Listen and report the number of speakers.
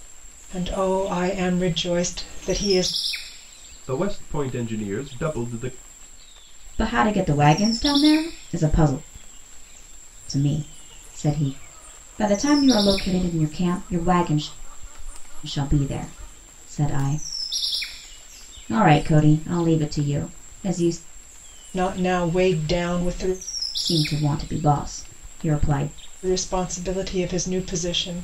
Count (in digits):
3